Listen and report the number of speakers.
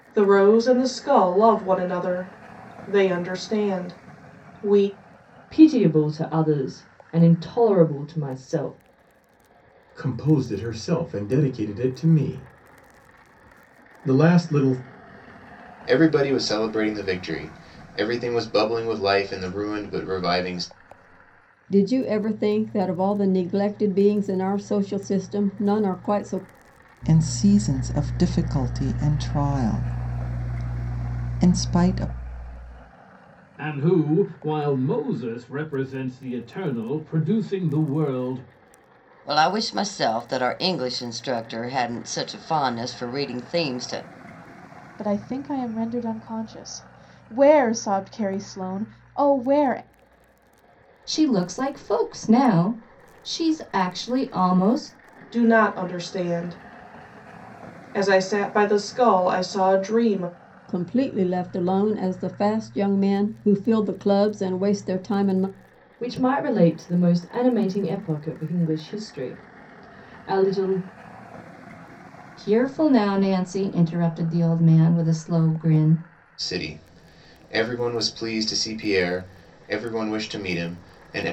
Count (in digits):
10